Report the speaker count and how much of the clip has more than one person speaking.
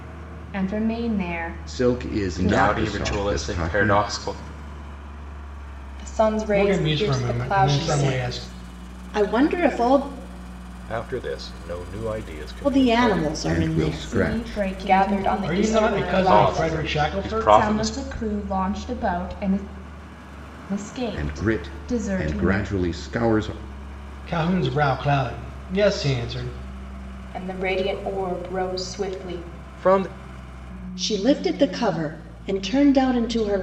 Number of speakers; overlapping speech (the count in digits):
7, about 38%